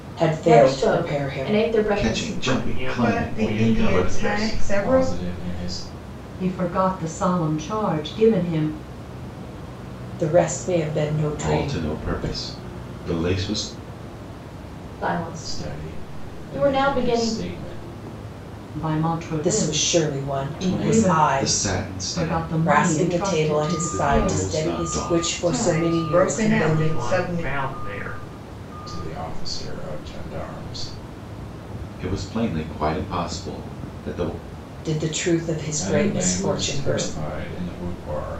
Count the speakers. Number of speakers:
seven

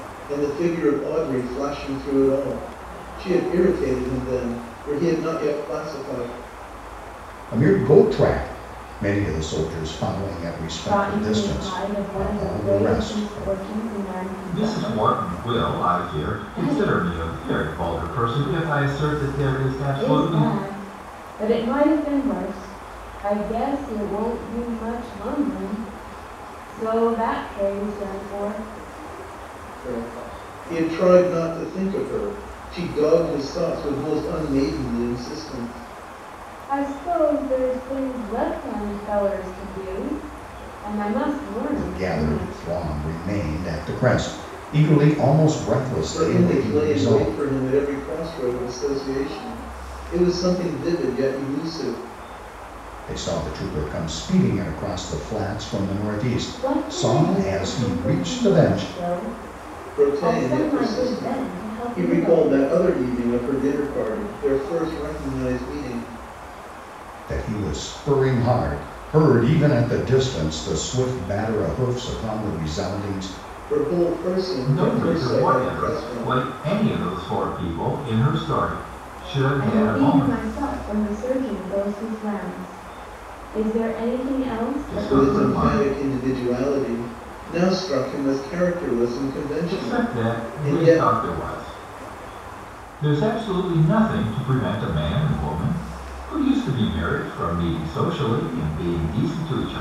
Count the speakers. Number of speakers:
four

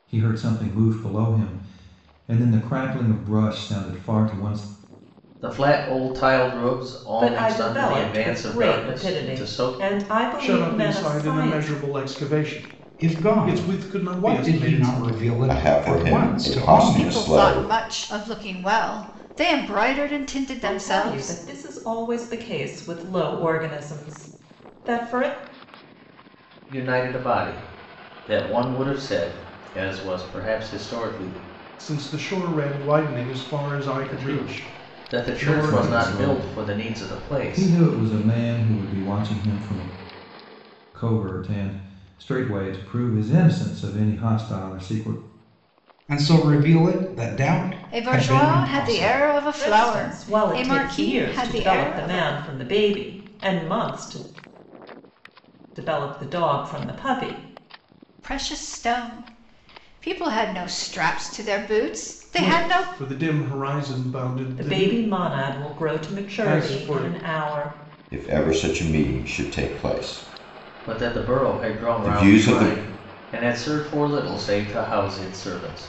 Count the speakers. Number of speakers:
seven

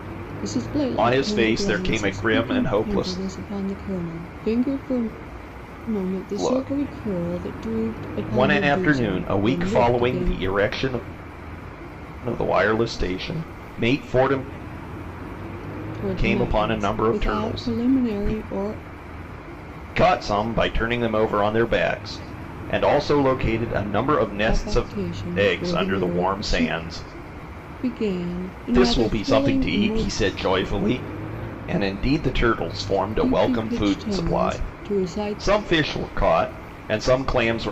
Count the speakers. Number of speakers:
two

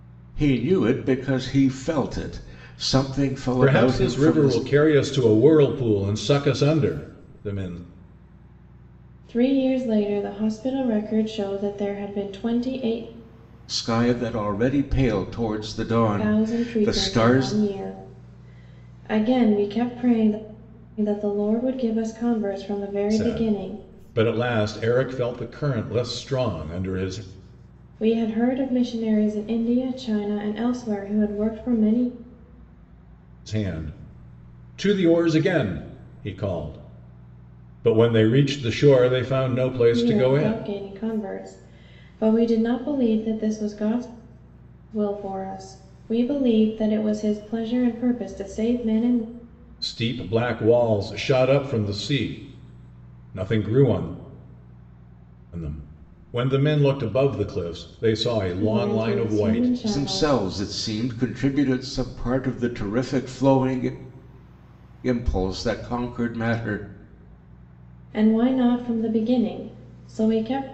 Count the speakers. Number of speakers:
three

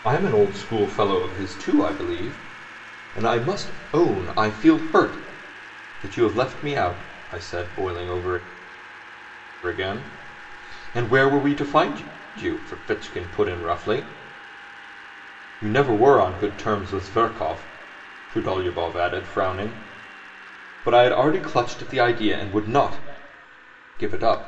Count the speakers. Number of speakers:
one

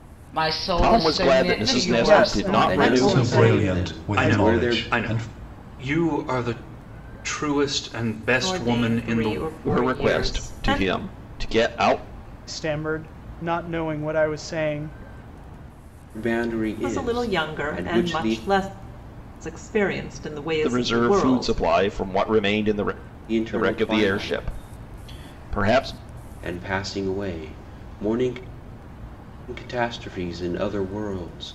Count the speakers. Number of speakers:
seven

